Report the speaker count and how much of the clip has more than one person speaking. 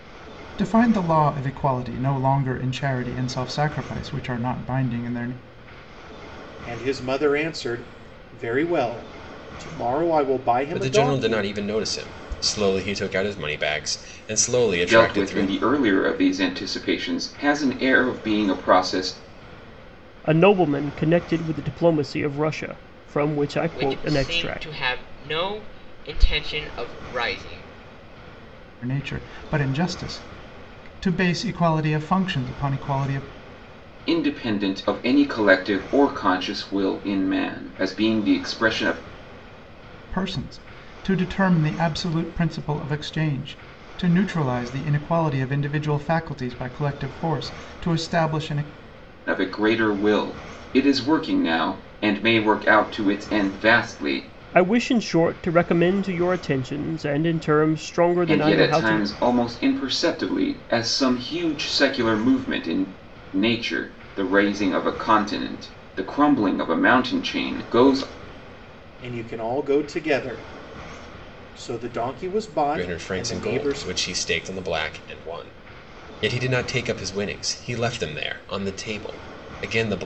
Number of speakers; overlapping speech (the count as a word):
six, about 6%